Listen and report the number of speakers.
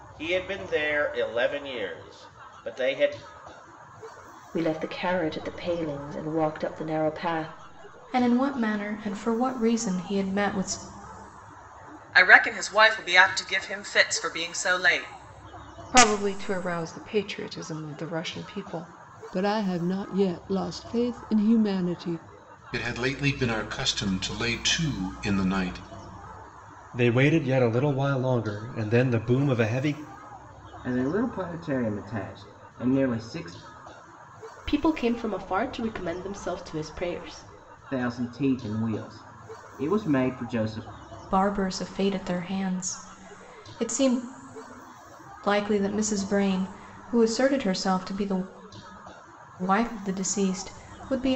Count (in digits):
10